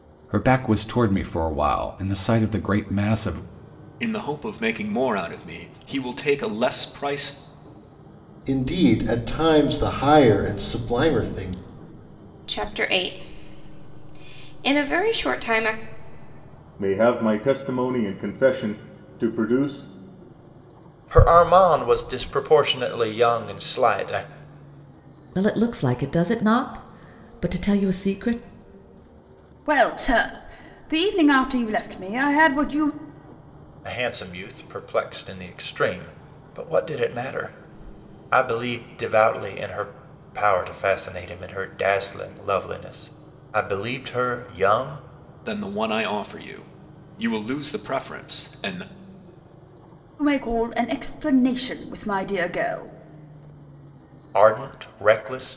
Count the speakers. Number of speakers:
eight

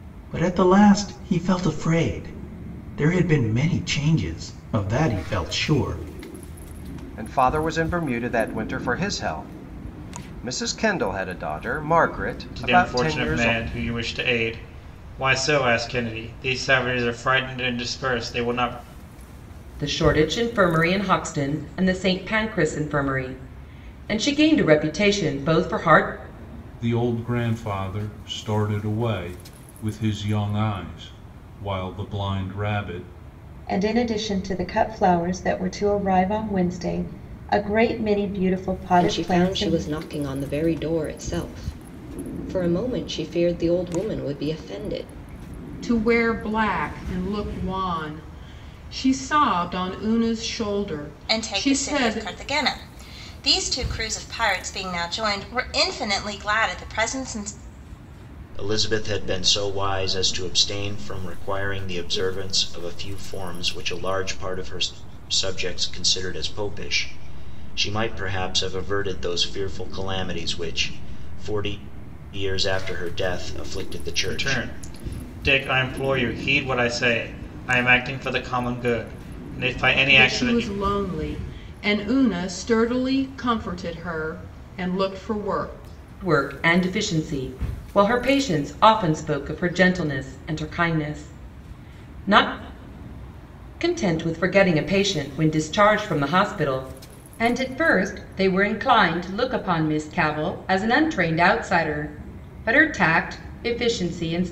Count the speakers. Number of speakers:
ten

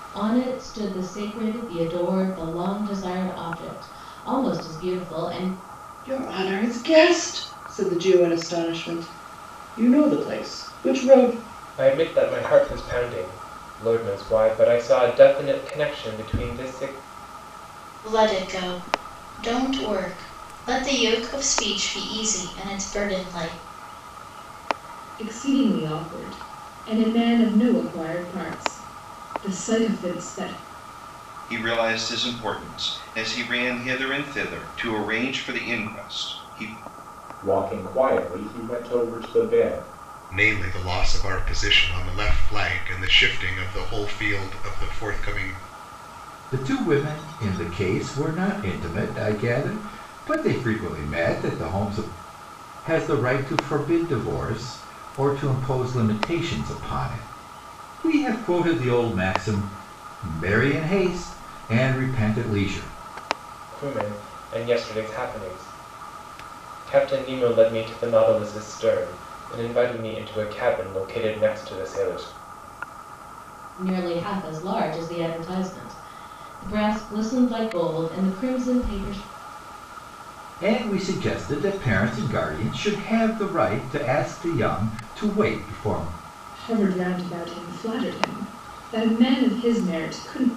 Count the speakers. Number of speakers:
nine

